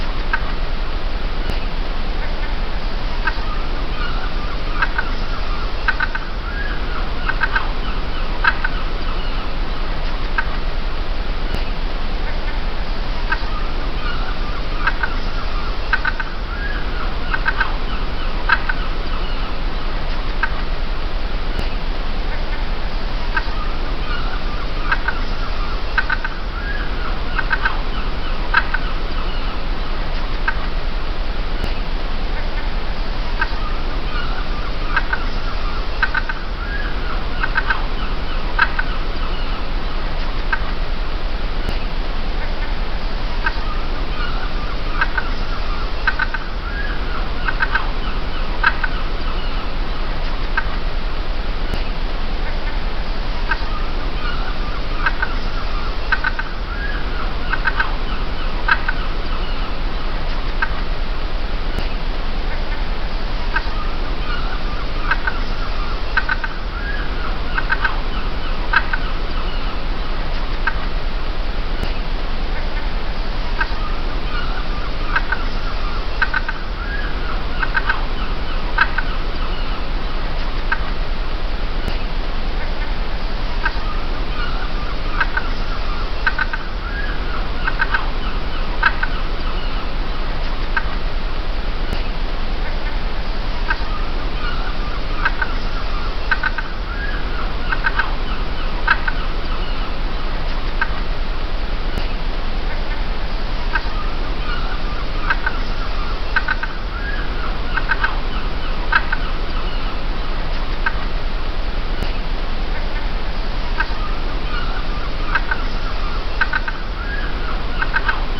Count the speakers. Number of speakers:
0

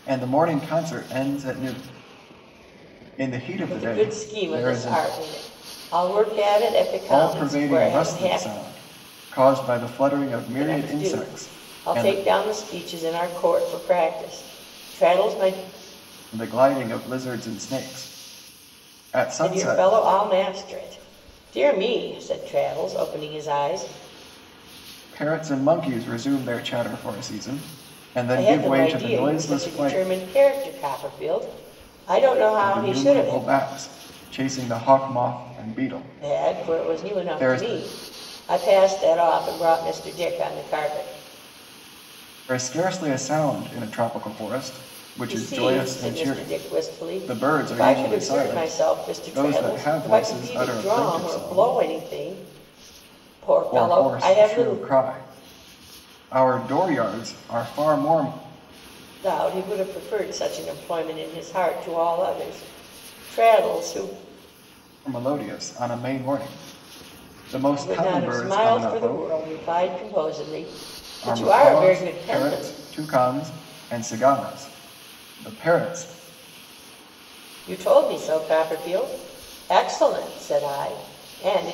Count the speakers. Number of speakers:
2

